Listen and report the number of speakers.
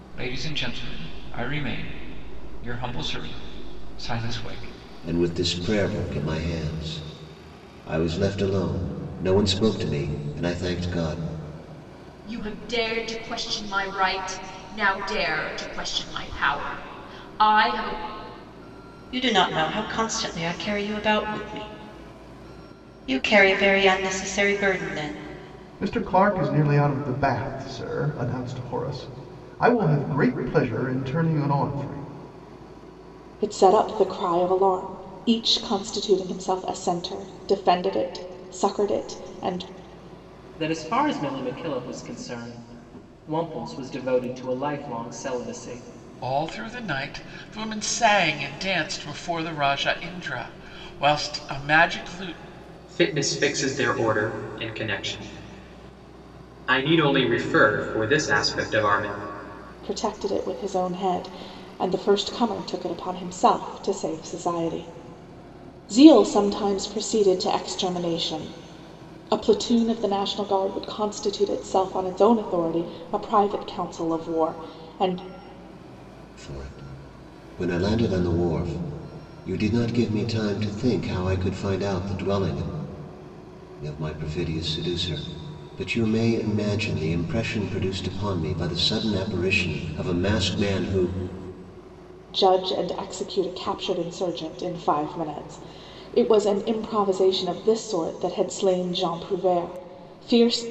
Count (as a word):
nine